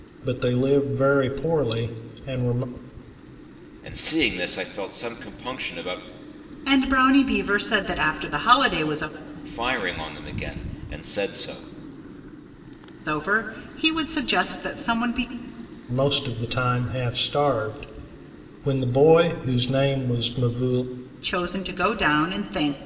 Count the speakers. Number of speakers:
3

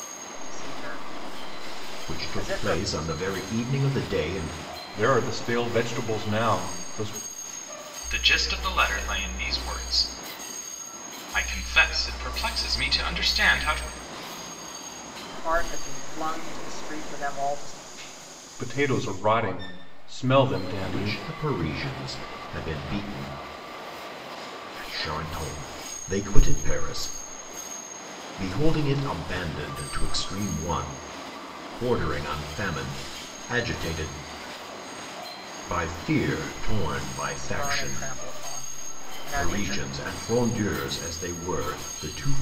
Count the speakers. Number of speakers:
4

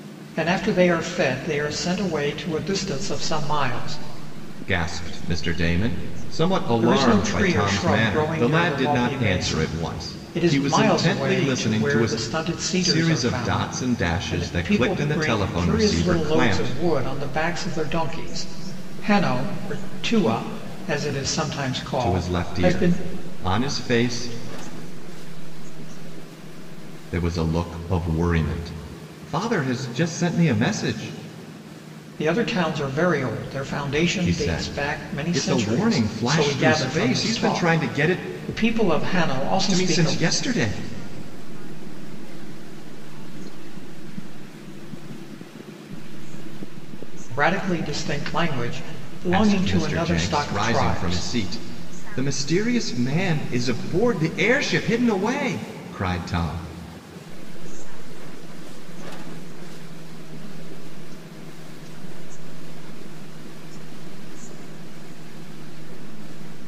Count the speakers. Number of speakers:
3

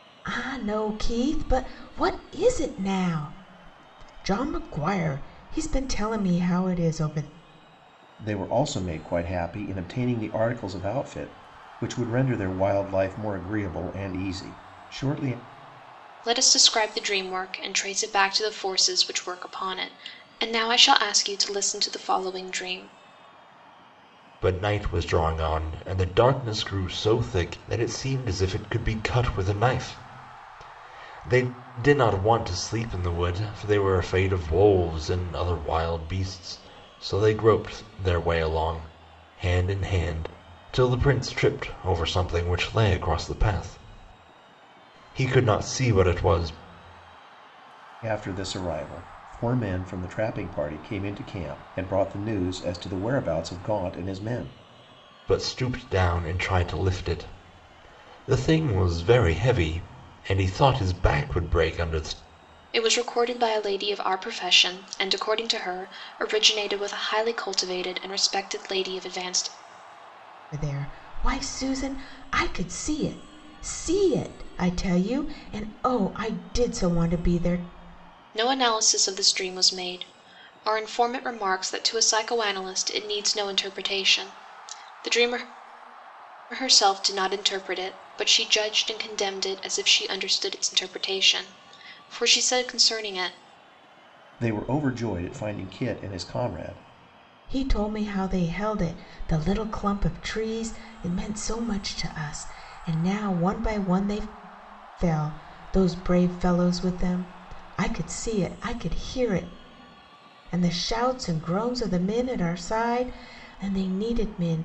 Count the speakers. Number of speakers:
4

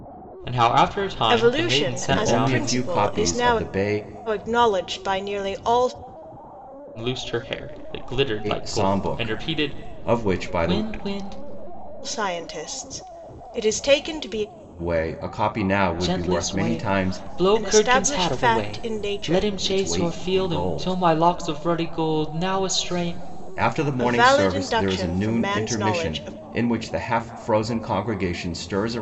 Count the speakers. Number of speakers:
3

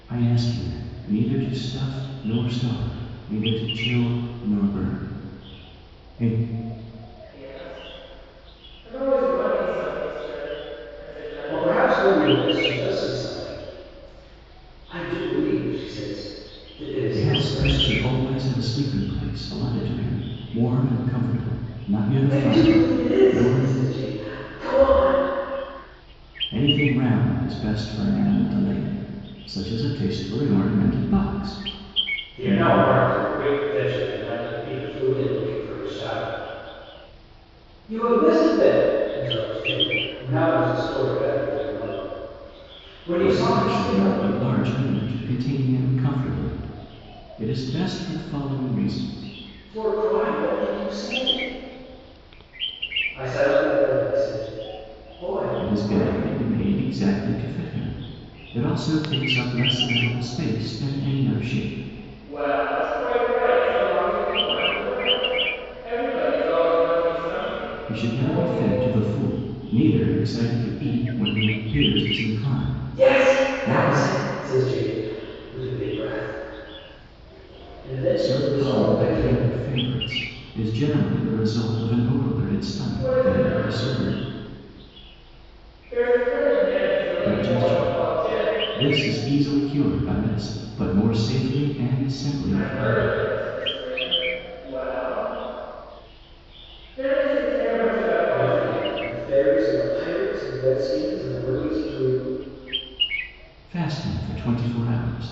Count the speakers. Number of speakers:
3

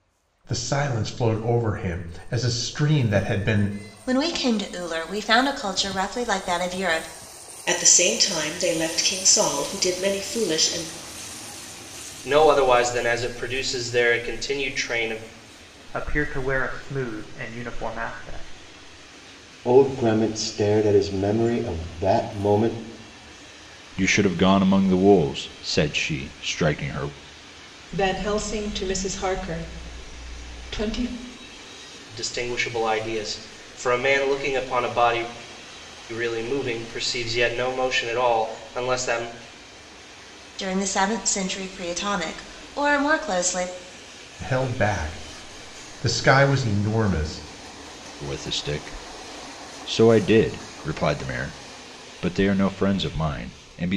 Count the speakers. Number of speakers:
8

